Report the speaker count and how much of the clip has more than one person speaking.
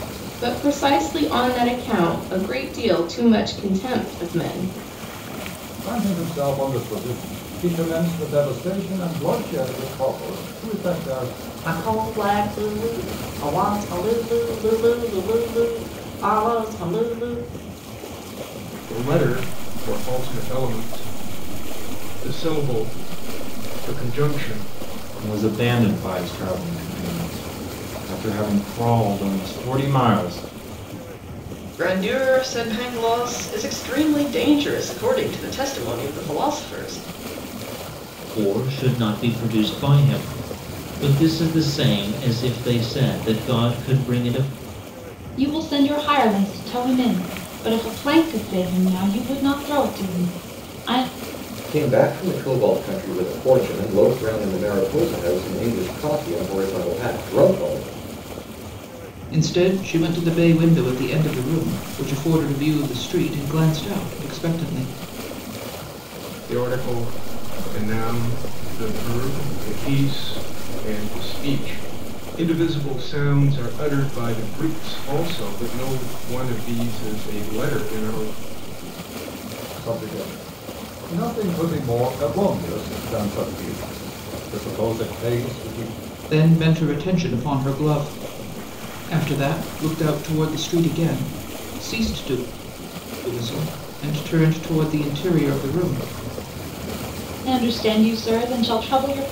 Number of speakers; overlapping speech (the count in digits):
10, no overlap